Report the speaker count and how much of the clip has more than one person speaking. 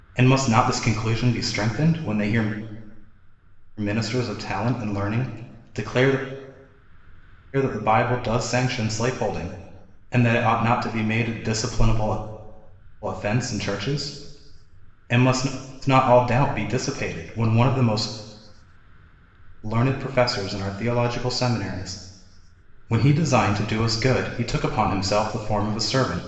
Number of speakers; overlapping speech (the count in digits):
1, no overlap